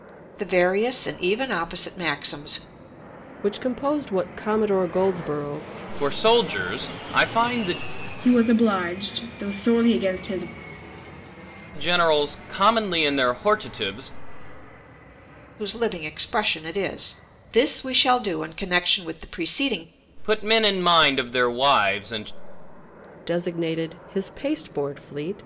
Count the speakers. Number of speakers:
4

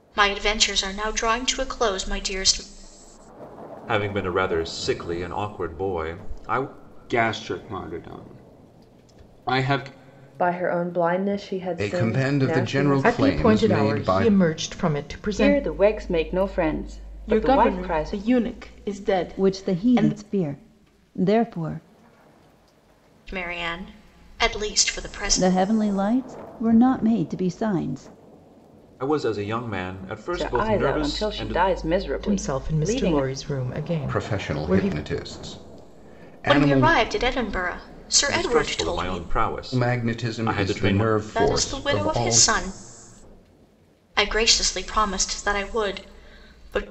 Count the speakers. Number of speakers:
9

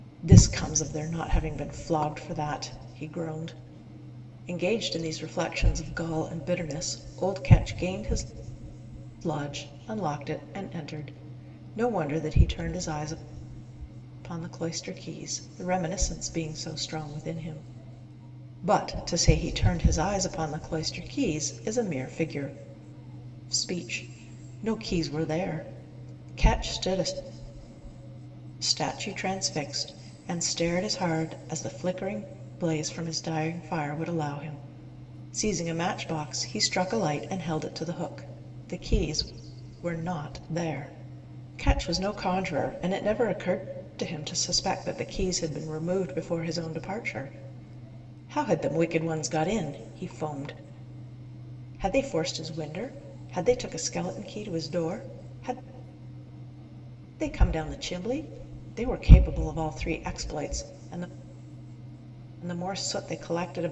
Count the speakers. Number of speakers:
1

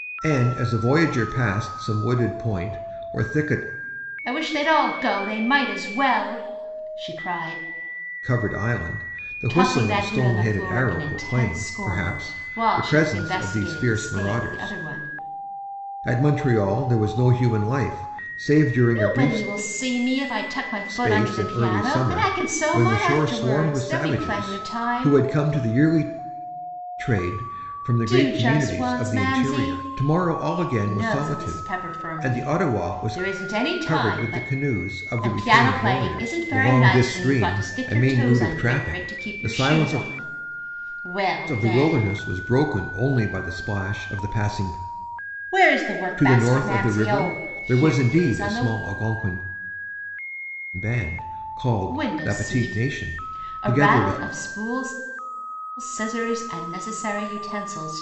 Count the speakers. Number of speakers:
2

